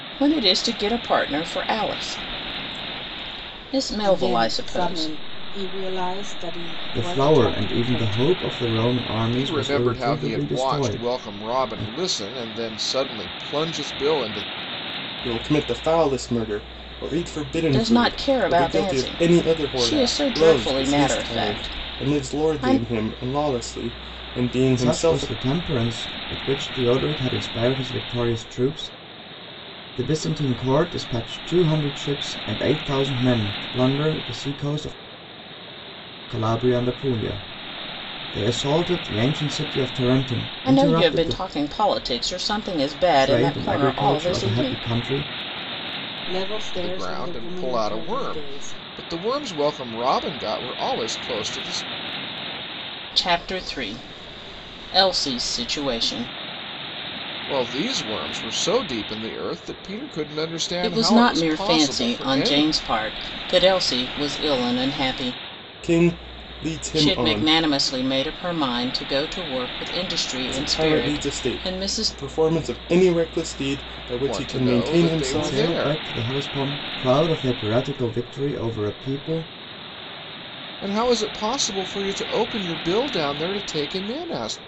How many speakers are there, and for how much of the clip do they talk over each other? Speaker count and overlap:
5, about 26%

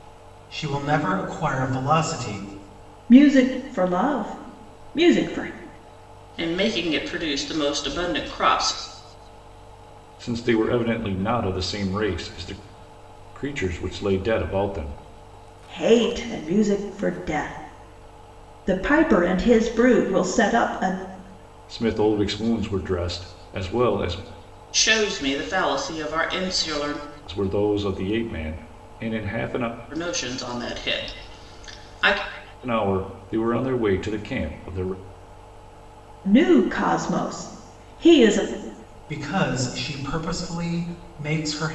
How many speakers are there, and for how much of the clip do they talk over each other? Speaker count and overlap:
4, no overlap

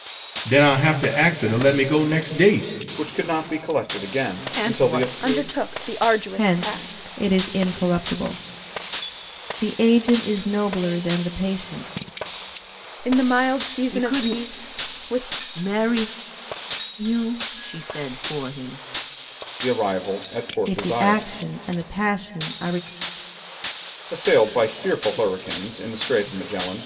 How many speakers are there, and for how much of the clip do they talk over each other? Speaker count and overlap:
5, about 16%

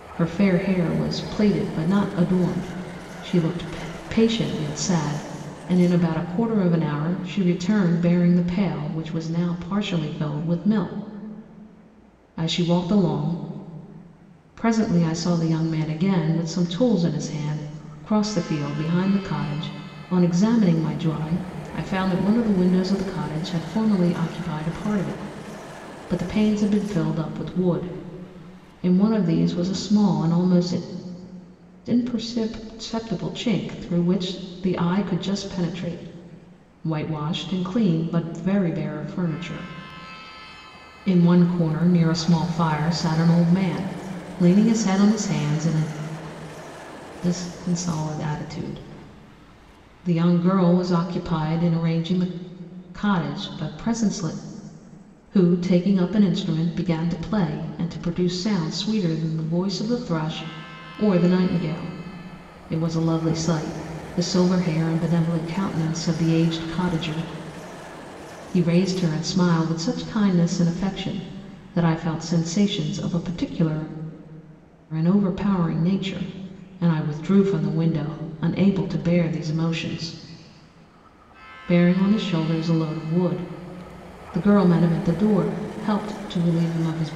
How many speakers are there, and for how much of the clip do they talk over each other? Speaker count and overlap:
1, no overlap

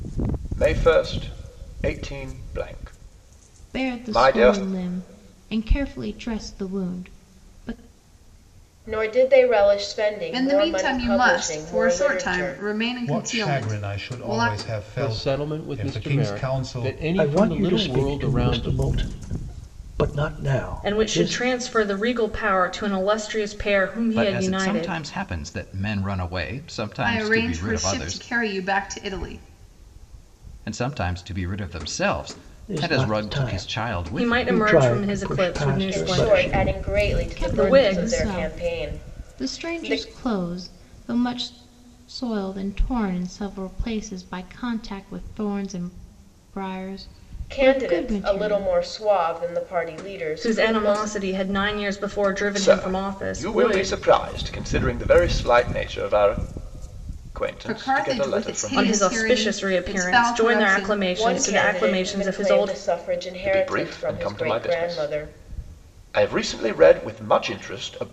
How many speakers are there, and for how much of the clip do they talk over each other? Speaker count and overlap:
9, about 43%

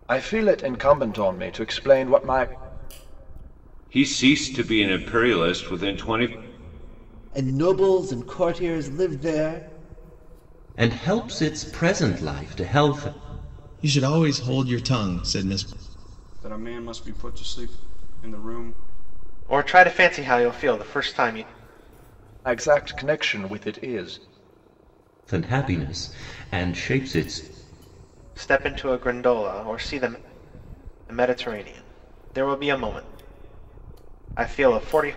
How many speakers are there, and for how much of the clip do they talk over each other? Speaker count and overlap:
7, no overlap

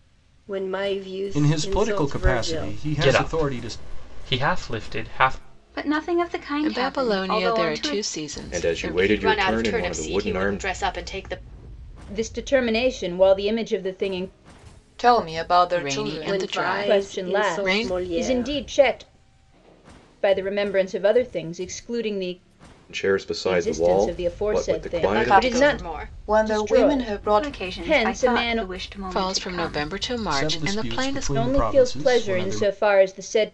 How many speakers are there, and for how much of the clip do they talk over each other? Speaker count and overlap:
9, about 51%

